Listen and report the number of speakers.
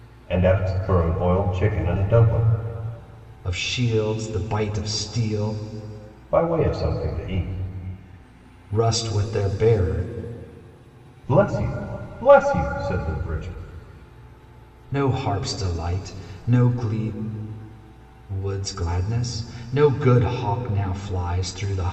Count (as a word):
two